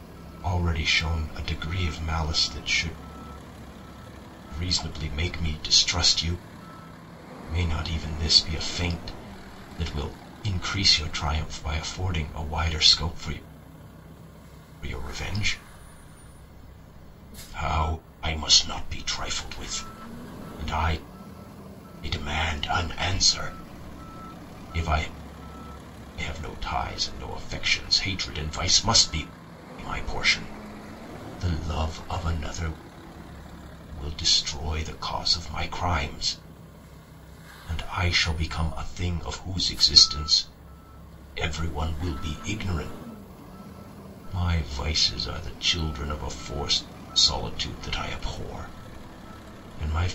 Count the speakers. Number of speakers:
one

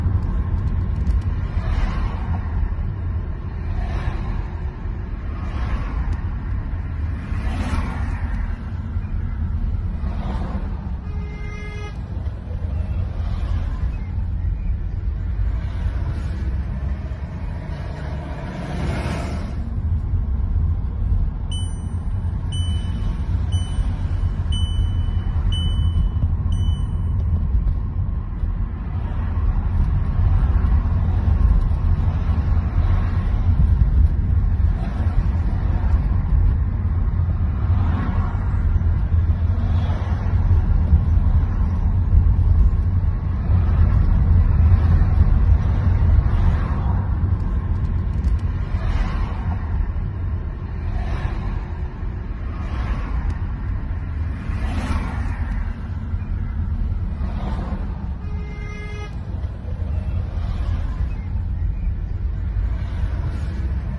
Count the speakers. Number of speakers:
zero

